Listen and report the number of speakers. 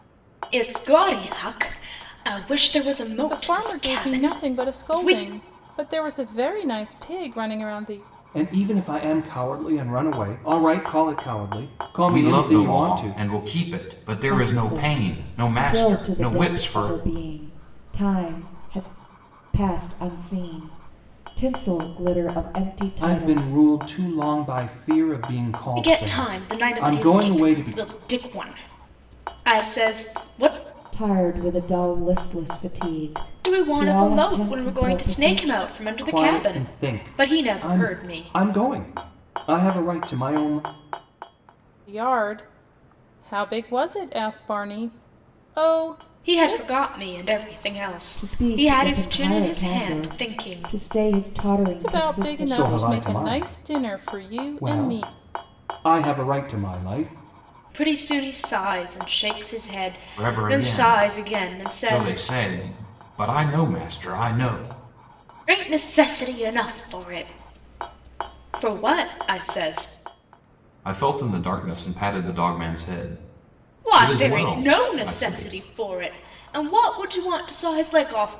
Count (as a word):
five